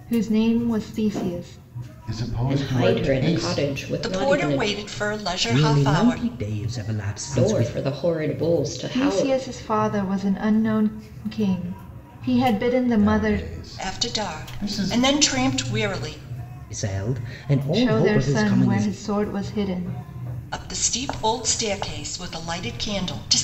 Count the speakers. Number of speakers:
5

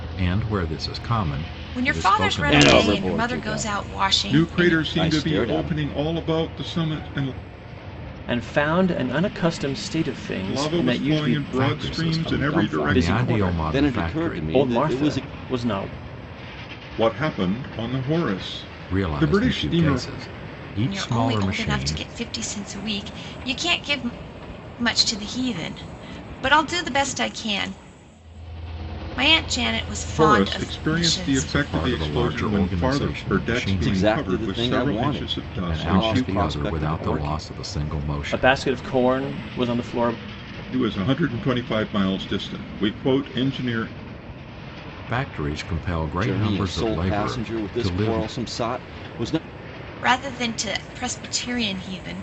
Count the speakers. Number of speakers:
5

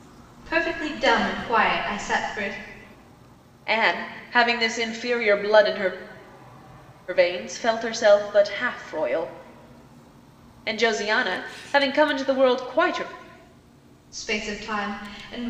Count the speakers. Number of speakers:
2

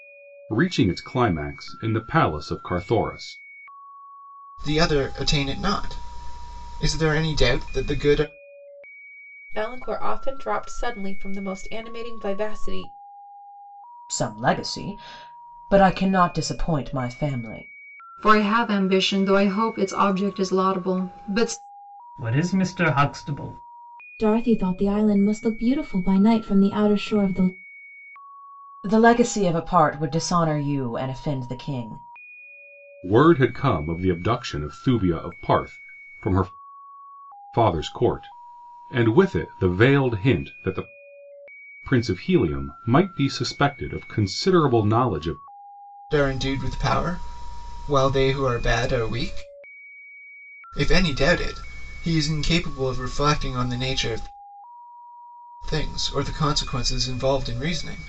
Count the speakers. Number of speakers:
7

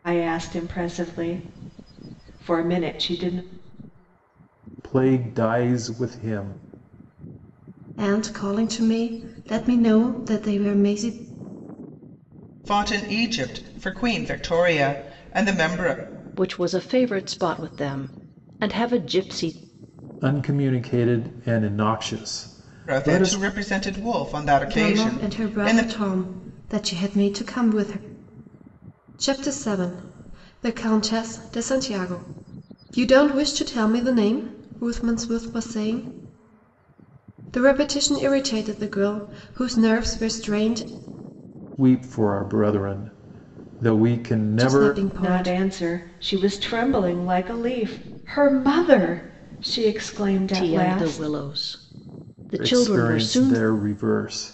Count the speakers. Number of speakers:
5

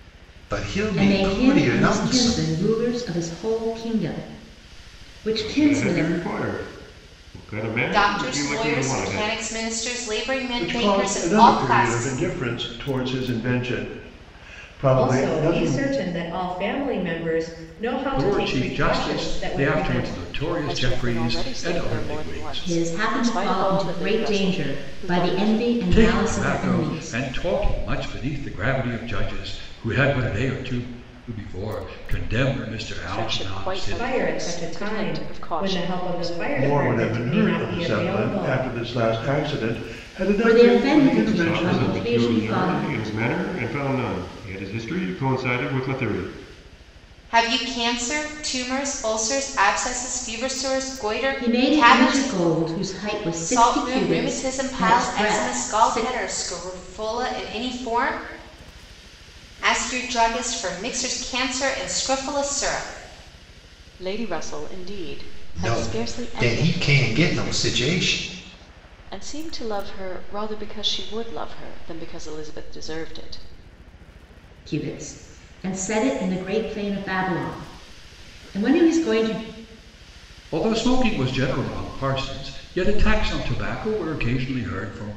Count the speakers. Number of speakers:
8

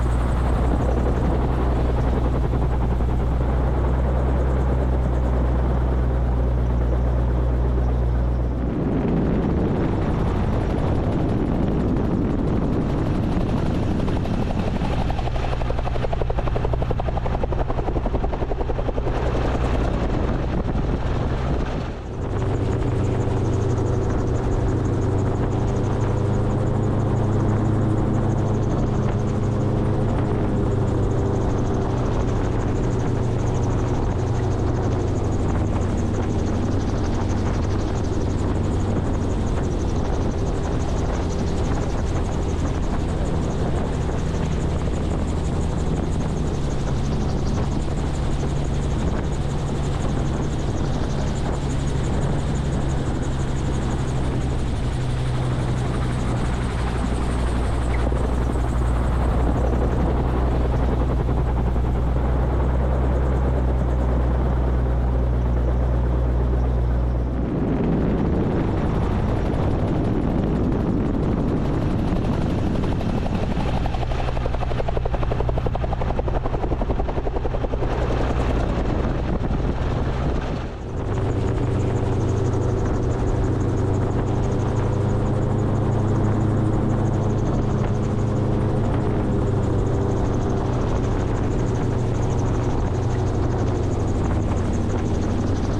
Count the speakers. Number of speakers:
0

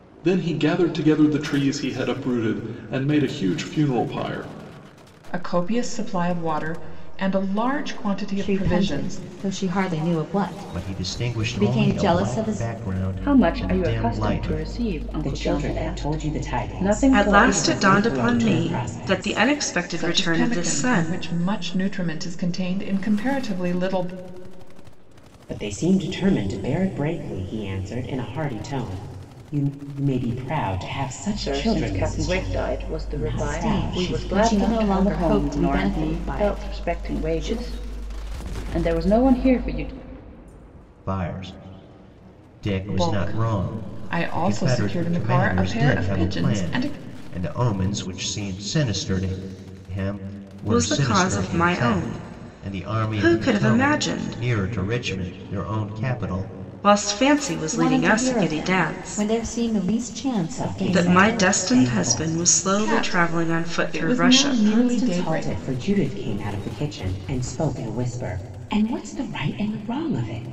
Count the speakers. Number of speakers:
7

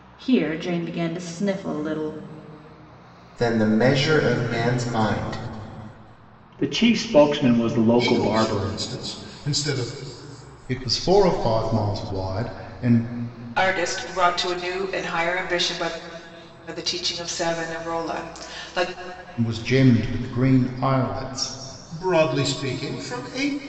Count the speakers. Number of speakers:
6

